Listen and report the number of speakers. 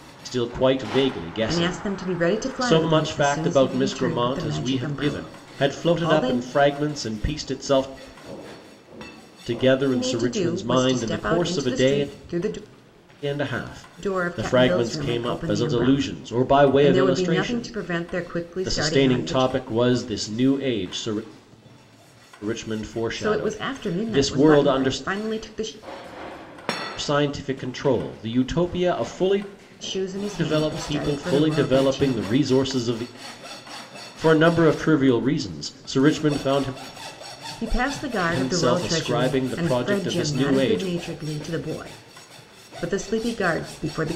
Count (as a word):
two